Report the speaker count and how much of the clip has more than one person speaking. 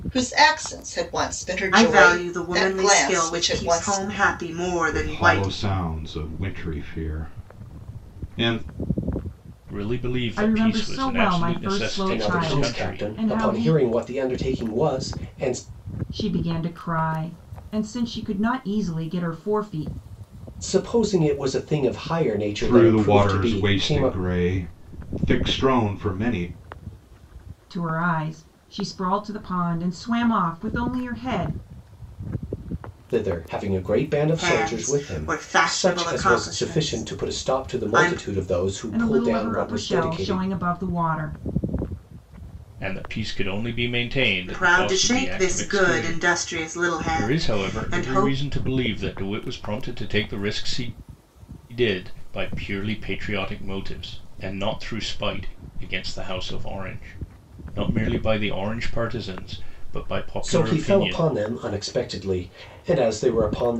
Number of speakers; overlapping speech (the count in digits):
6, about 28%